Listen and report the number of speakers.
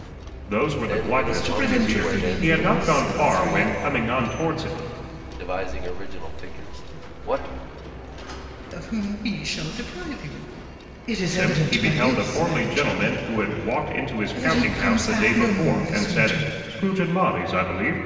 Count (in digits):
3